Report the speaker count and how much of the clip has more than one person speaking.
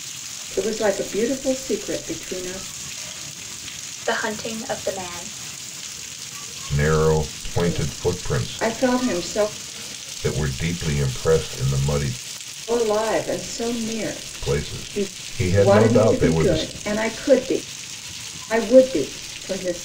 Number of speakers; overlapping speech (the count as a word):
three, about 15%